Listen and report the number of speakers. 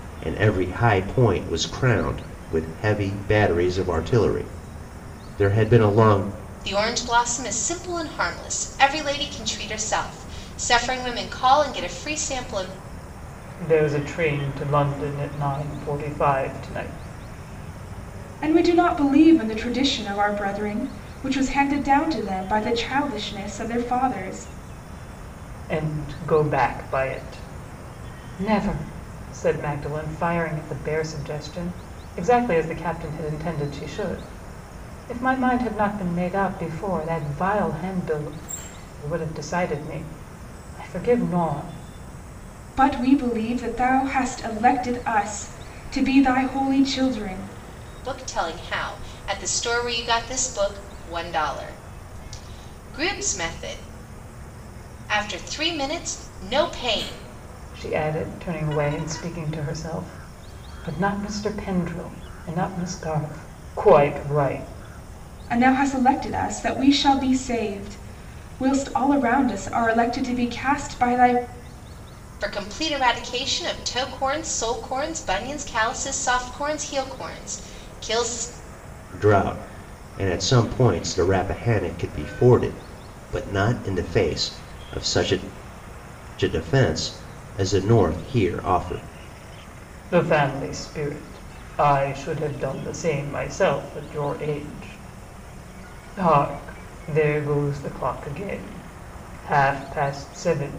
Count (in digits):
4